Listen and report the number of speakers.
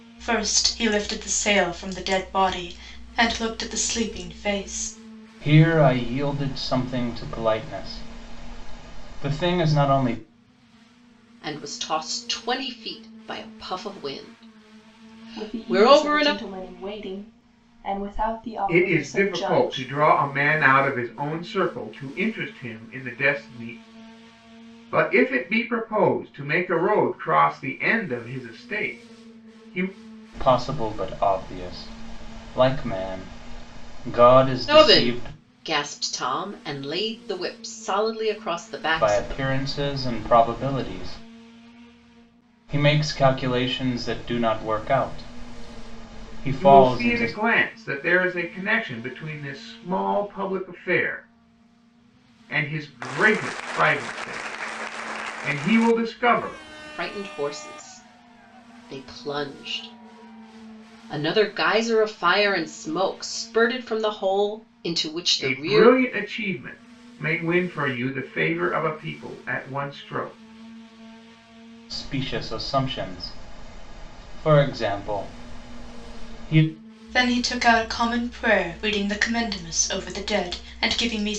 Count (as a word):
five